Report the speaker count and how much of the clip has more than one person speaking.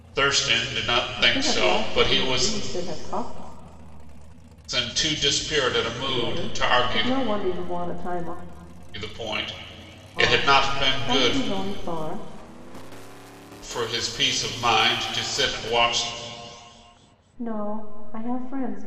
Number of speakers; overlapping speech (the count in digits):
2, about 20%